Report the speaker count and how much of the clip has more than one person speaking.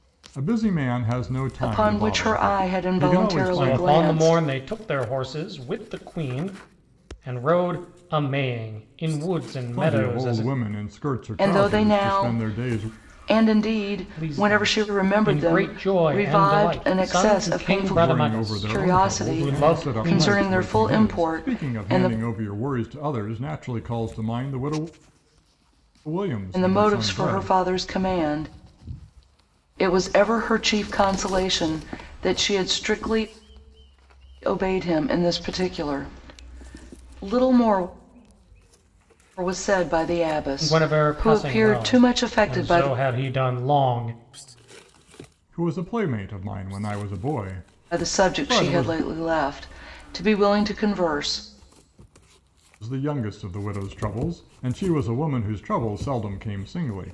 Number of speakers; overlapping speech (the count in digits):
3, about 31%